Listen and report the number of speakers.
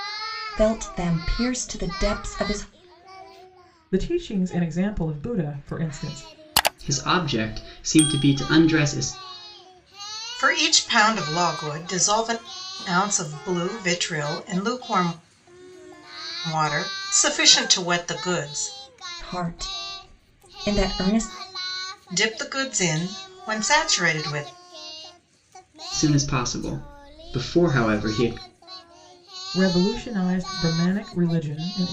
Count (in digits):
4